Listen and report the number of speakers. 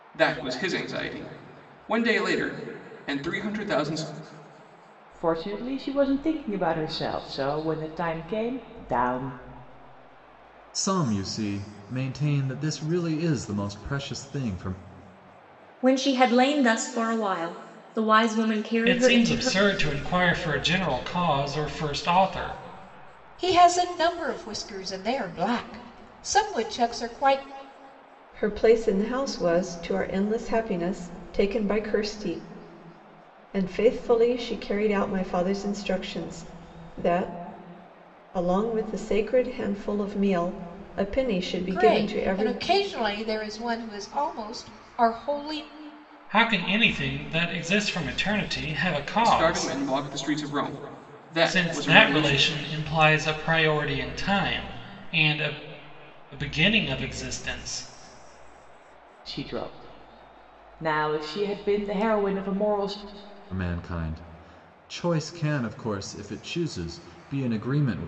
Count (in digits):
7